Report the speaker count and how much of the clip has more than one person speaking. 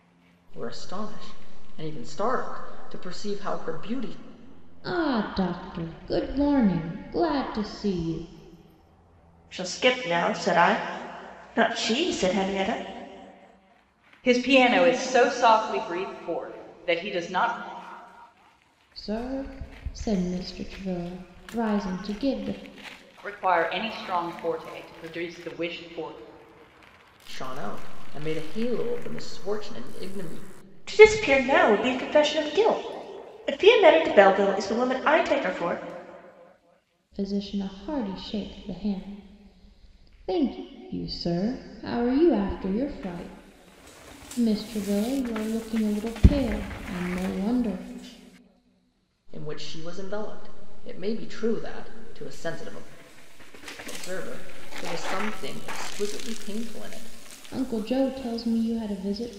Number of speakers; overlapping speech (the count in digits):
4, no overlap